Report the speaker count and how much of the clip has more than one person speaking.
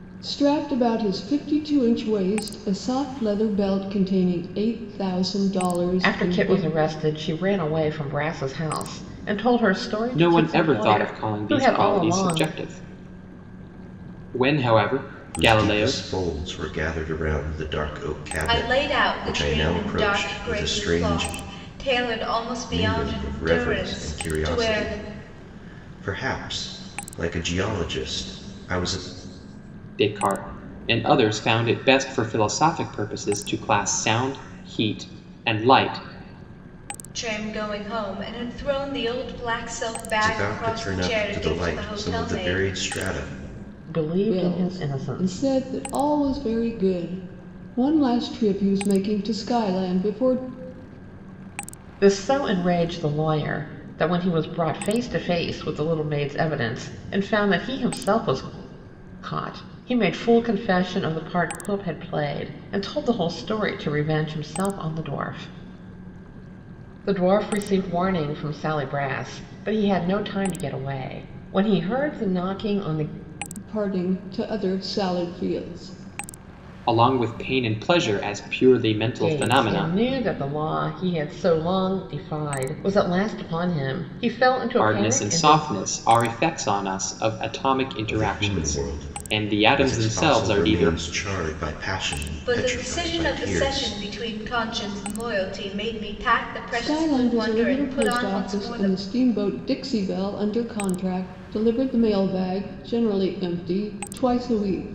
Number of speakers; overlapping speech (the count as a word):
five, about 20%